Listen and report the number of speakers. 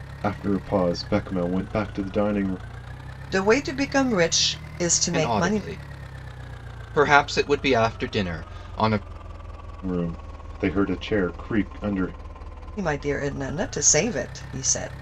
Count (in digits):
3